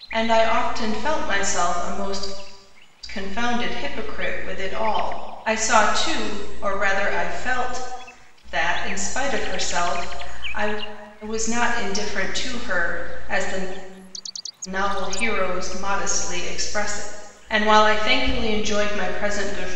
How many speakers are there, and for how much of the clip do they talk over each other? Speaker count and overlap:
1, no overlap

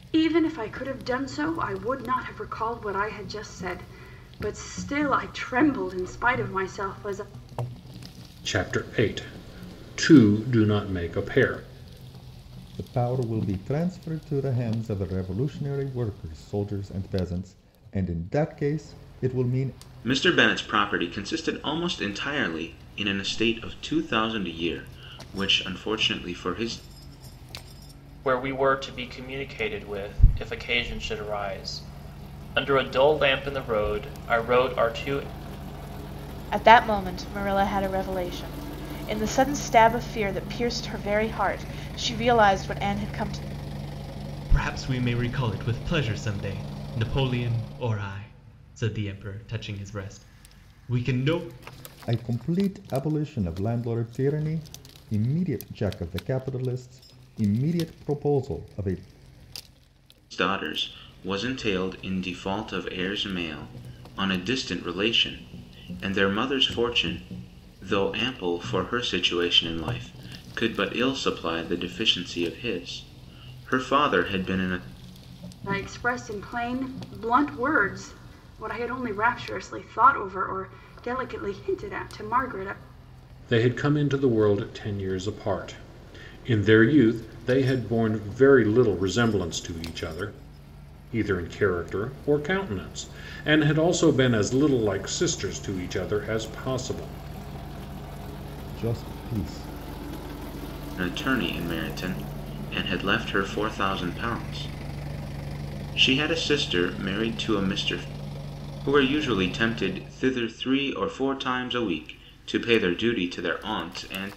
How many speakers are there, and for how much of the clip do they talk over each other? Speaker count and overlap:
7, no overlap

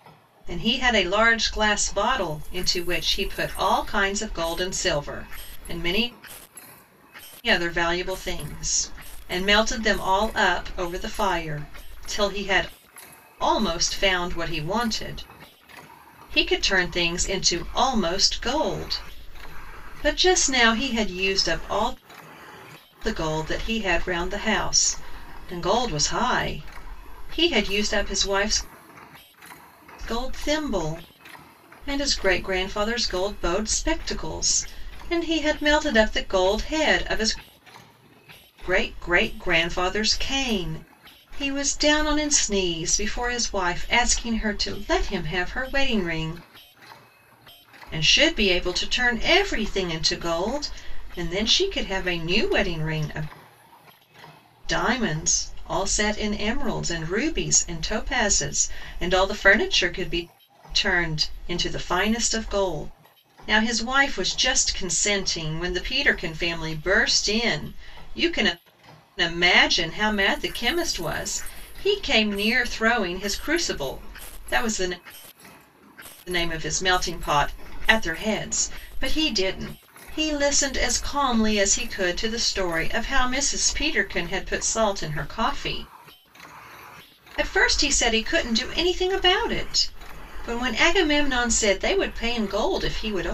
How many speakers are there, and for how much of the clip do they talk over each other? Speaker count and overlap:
1, no overlap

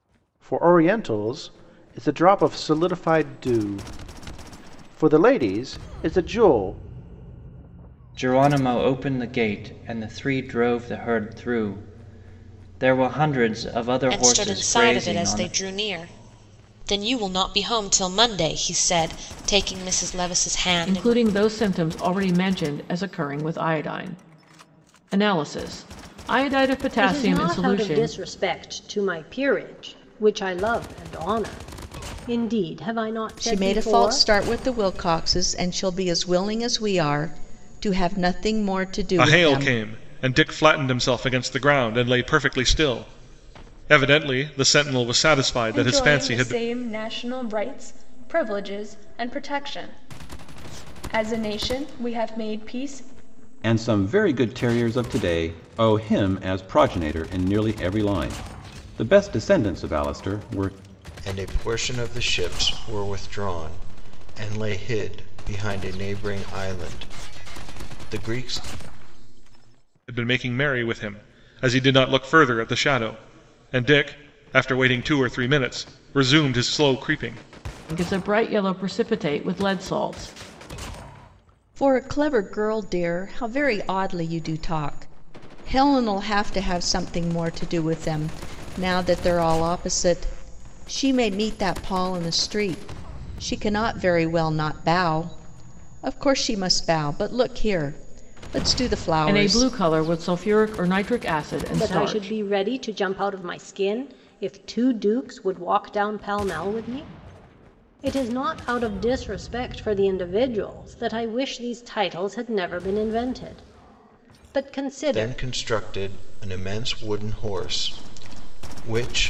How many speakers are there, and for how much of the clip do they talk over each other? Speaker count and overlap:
10, about 6%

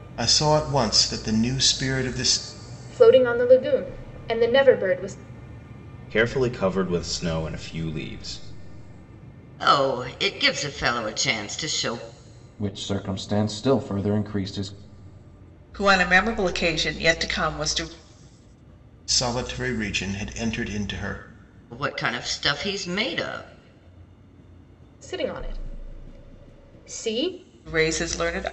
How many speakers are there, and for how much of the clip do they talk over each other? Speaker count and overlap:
6, no overlap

